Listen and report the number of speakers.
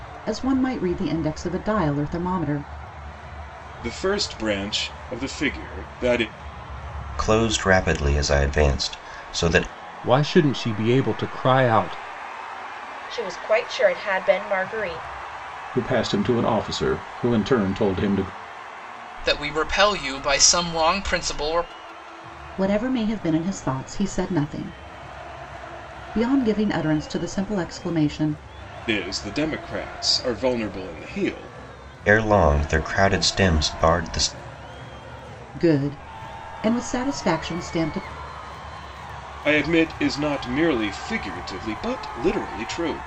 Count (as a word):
seven